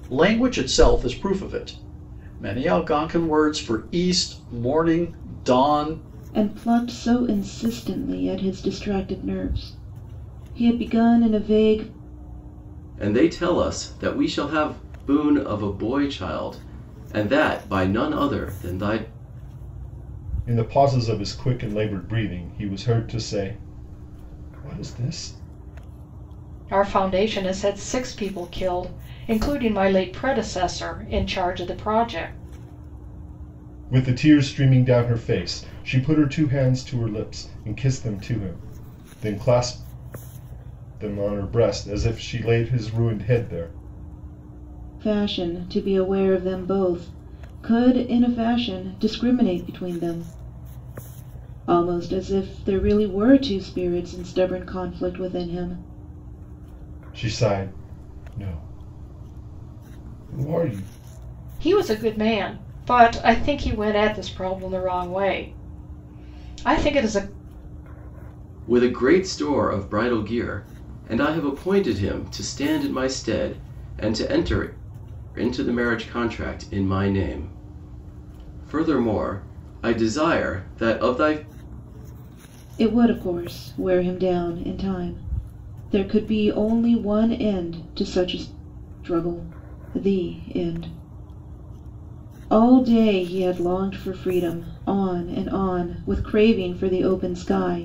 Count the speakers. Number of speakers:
5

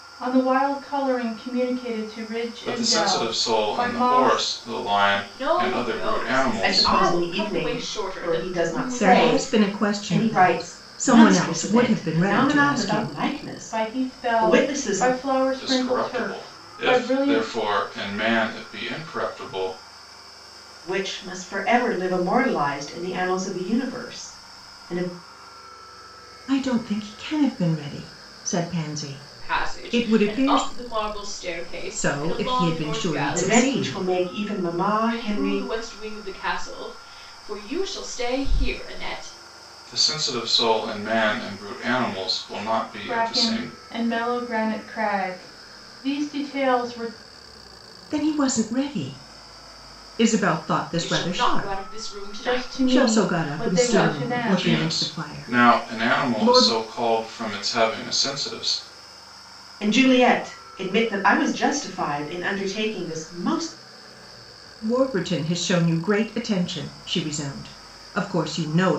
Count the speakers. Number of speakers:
5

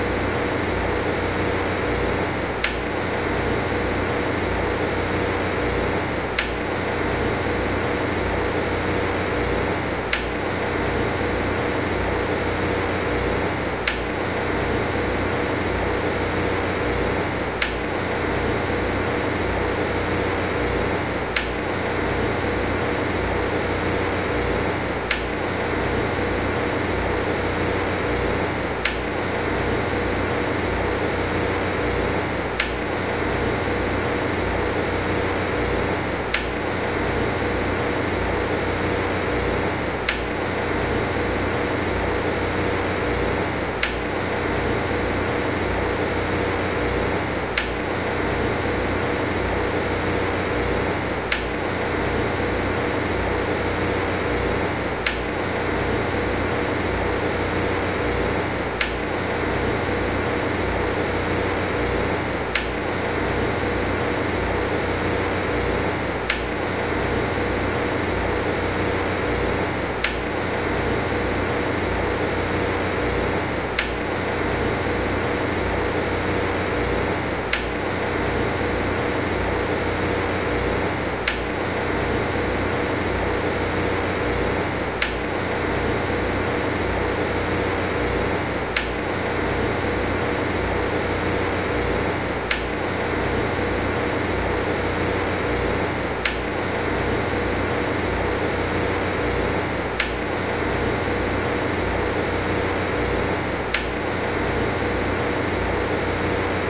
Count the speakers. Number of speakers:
0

